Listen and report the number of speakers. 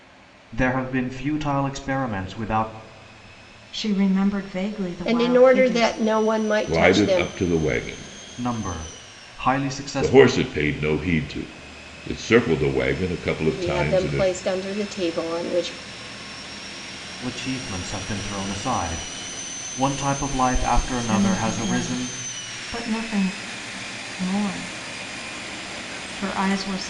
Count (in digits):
4